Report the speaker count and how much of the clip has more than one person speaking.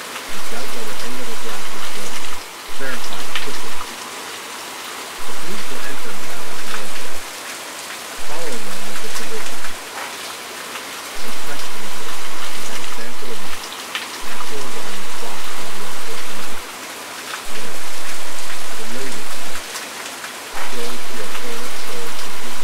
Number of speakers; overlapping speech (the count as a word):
one, no overlap